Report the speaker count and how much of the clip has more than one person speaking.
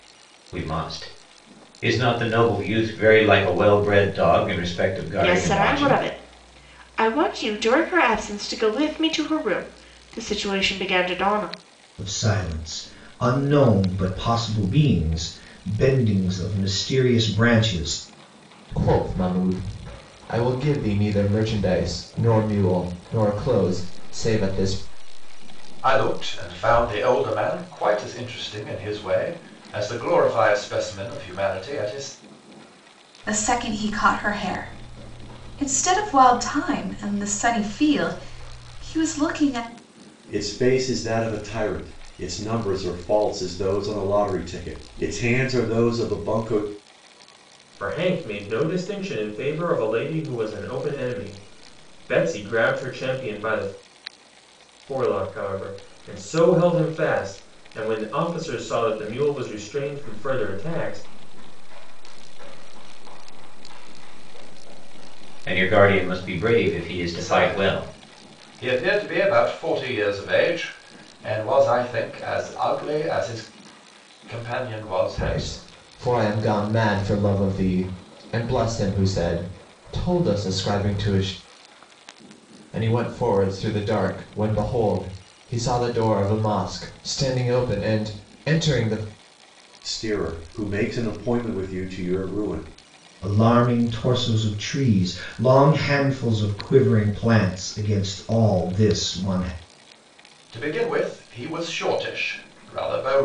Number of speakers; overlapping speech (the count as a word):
nine, about 6%